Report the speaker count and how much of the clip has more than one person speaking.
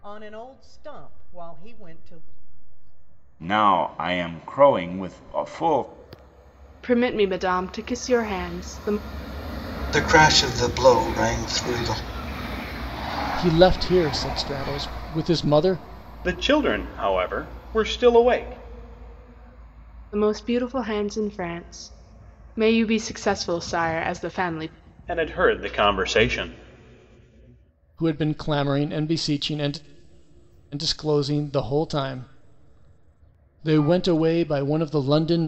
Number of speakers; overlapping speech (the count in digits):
6, no overlap